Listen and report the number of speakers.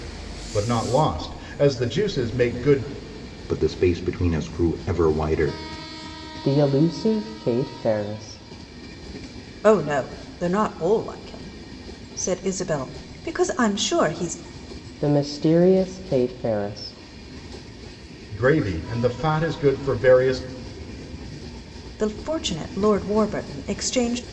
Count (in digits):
4